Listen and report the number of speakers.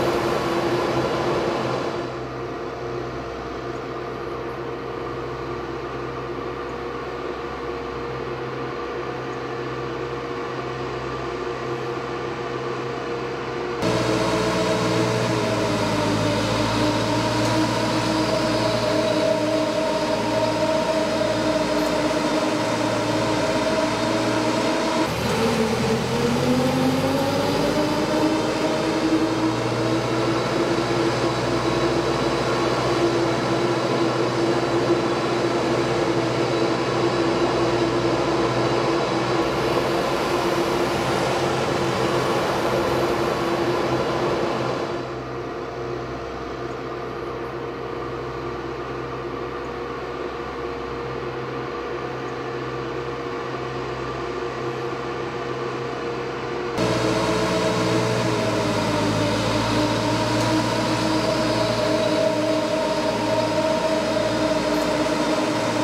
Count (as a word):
zero